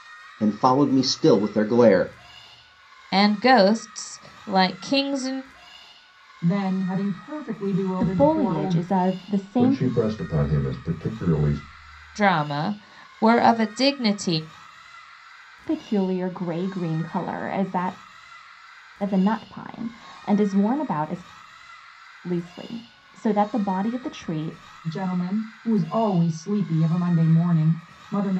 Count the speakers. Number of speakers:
five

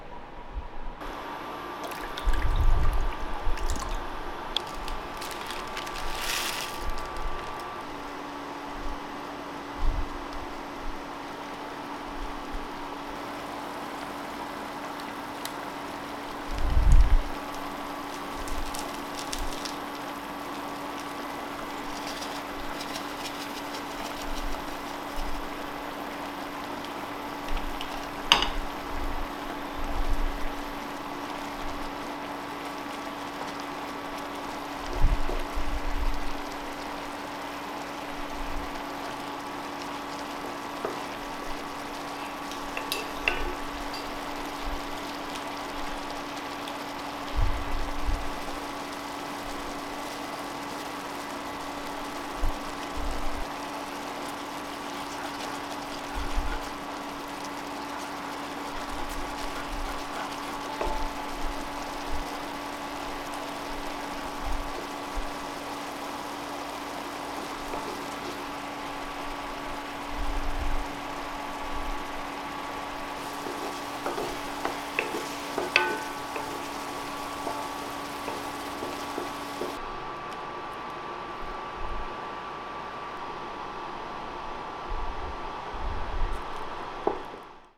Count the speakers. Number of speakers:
zero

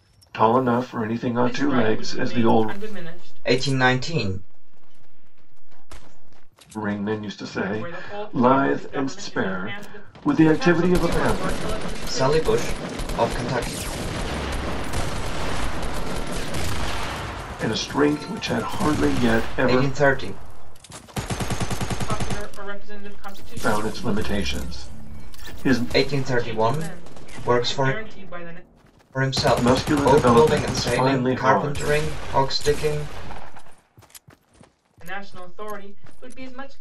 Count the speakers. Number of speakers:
four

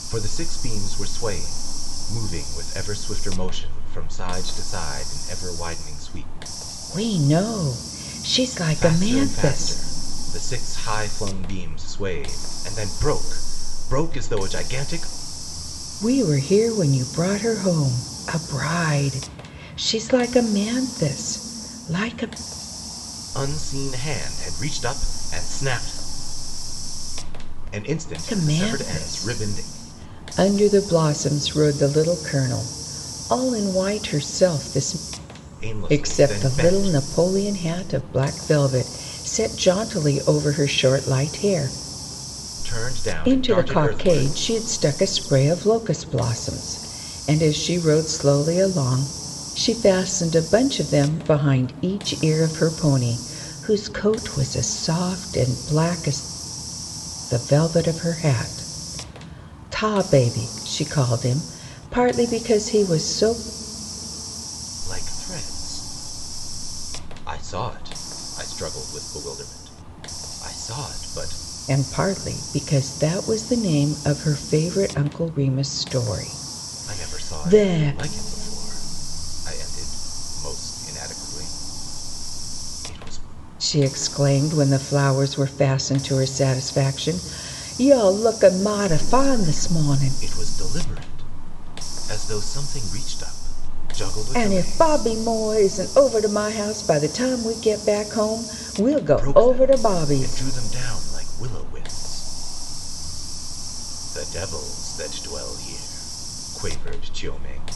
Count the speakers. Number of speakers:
two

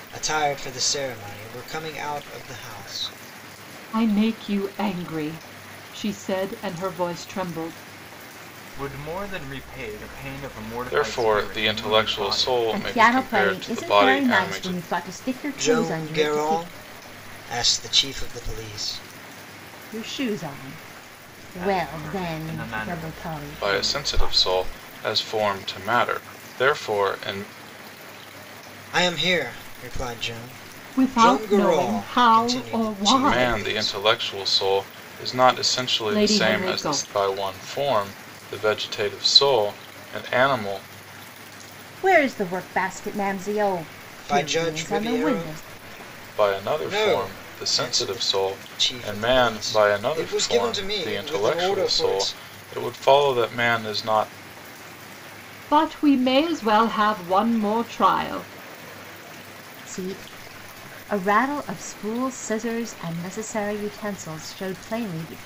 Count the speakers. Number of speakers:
five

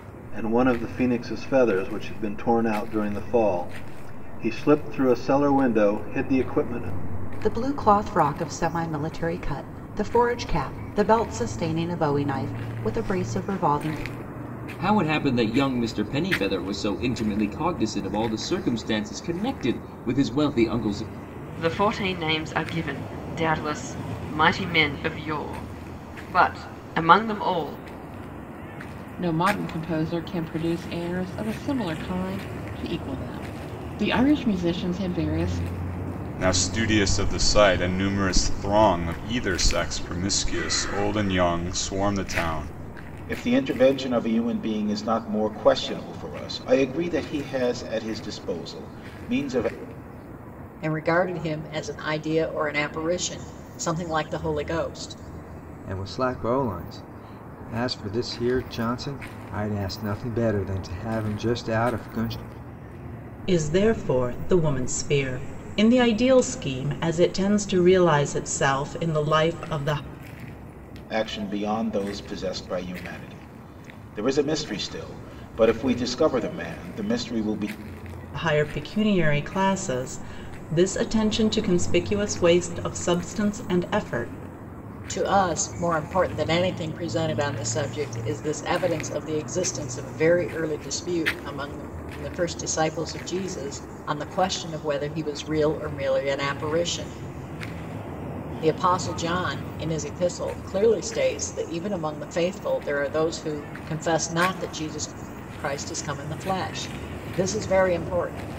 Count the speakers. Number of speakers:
ten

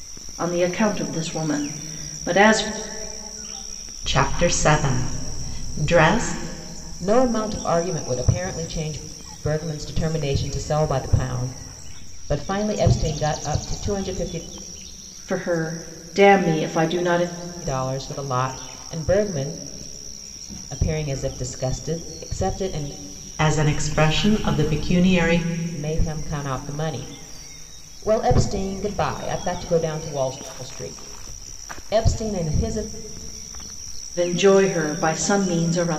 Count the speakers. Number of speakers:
three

